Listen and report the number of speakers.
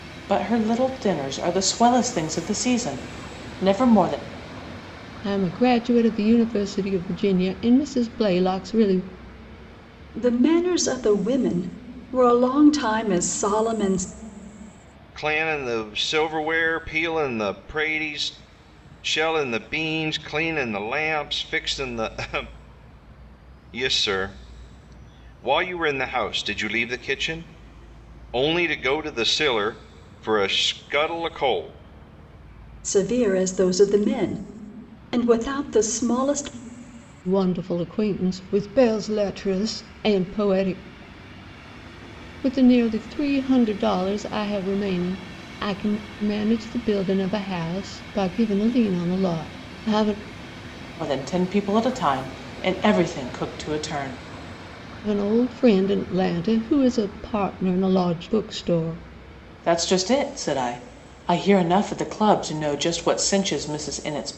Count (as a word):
four